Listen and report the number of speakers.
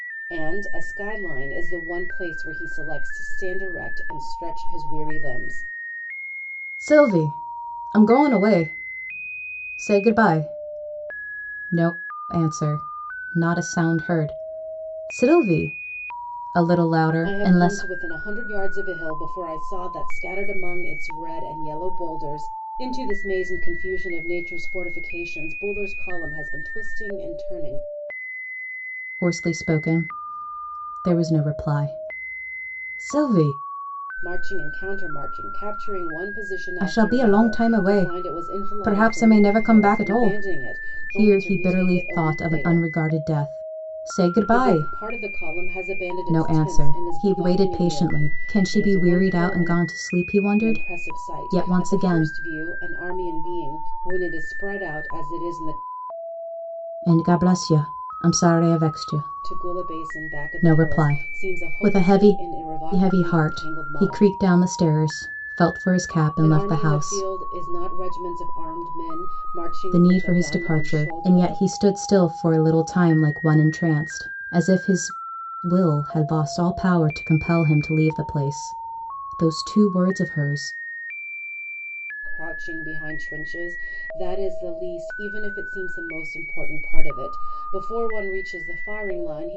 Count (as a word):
two